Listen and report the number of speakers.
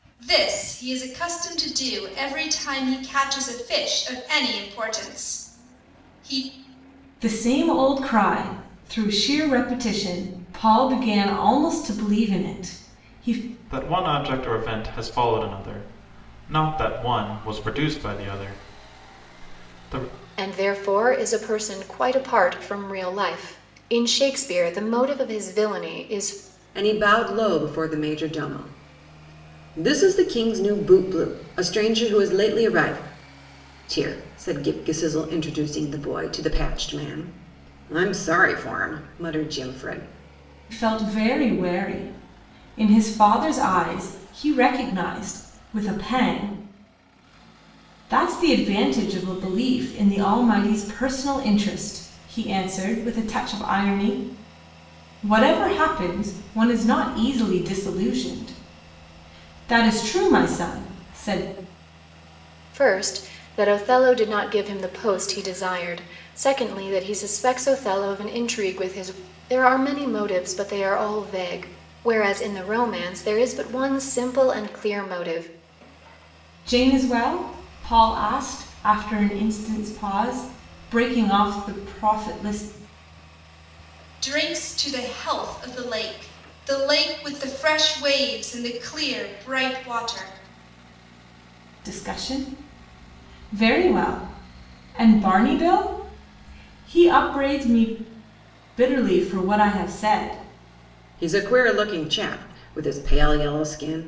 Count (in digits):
5